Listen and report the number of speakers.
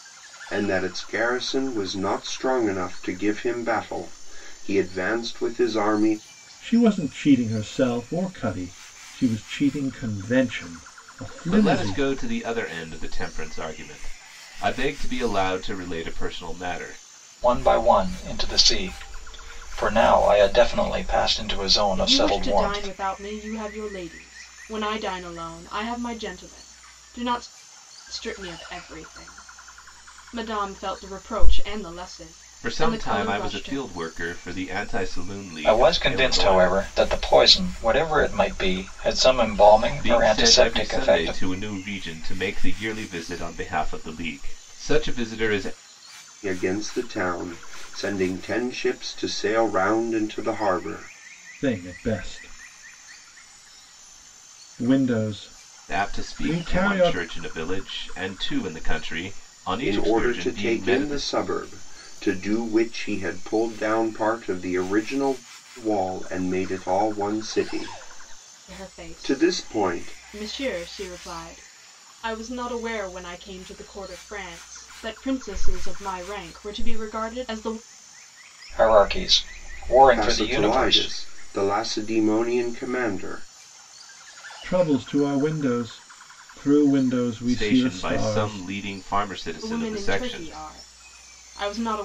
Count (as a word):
five